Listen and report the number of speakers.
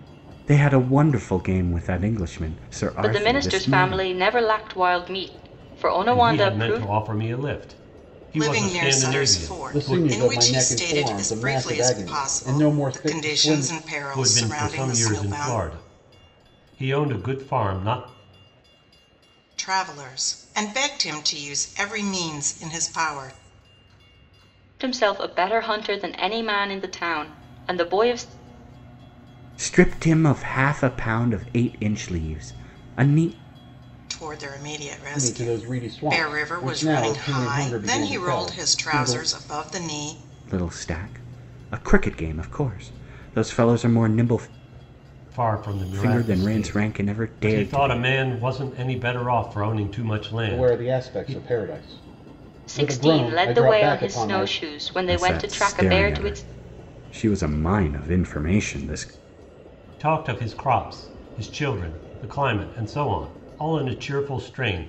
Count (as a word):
five